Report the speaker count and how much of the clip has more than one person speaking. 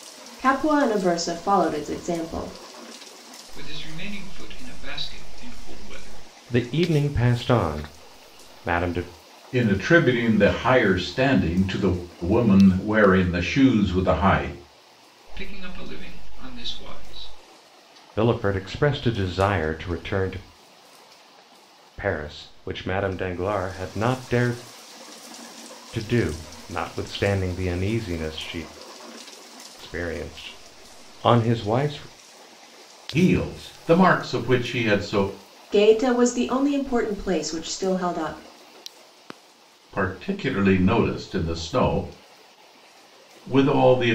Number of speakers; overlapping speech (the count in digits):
4, no overlap